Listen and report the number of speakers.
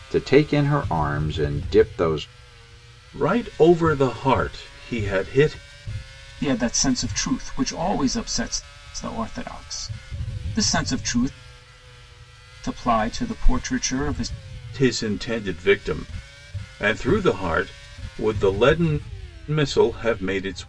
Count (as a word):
three